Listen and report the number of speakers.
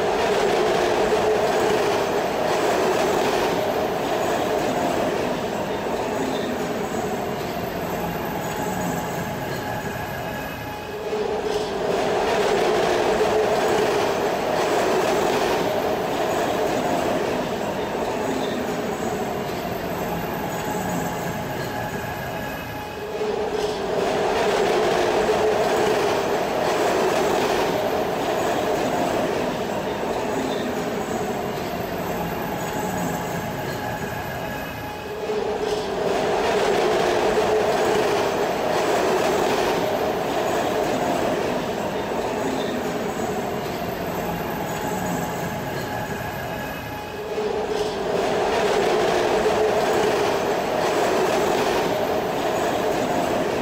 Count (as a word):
zero